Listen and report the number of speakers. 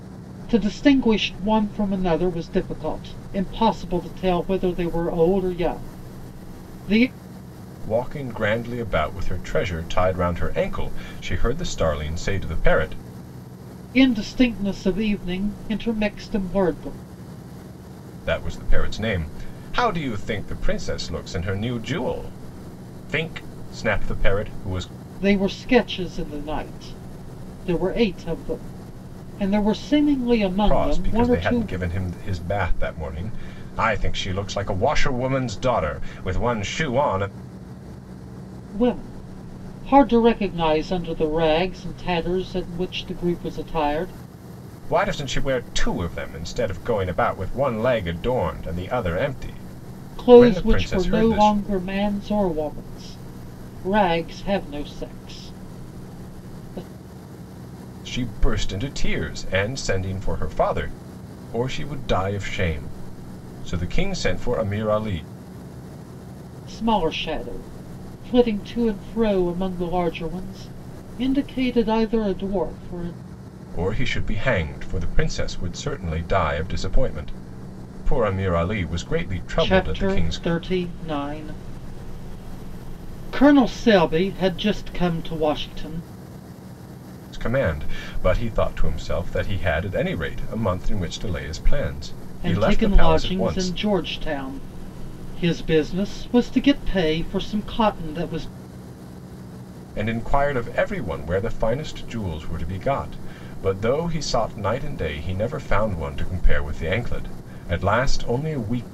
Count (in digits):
2